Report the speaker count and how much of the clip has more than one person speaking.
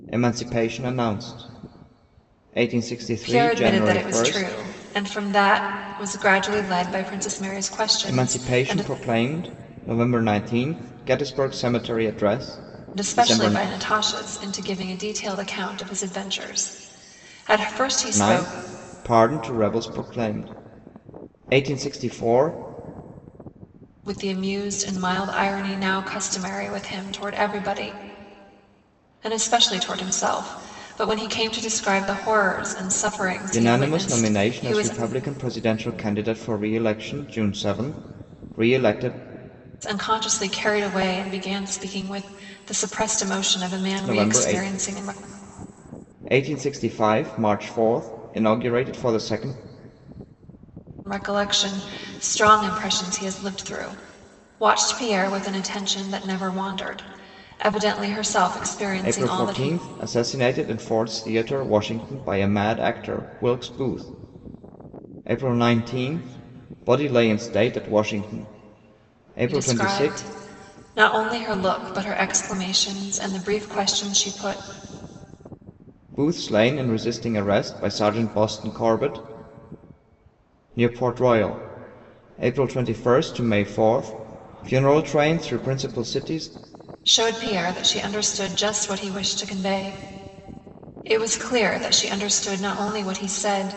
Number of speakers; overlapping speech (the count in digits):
2, about 8%